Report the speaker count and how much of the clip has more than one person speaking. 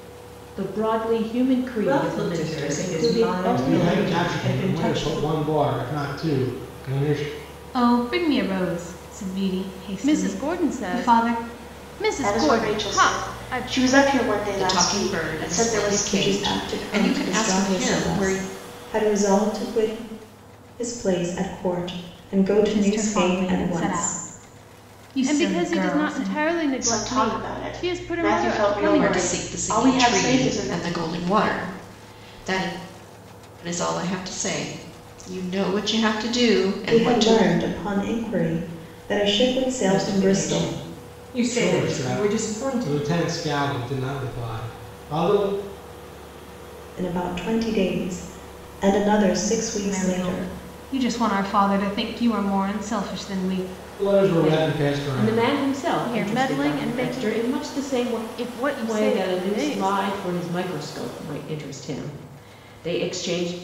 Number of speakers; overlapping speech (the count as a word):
eight, about 40%